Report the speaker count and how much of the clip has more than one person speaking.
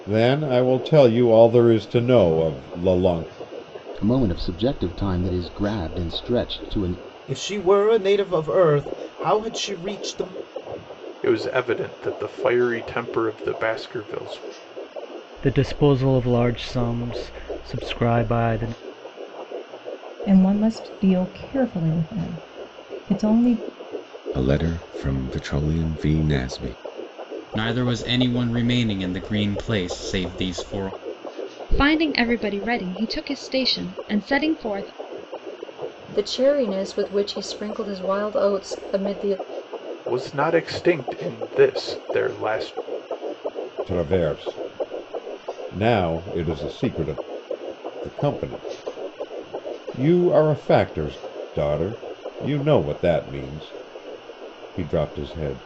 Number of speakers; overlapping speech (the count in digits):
10, no overlap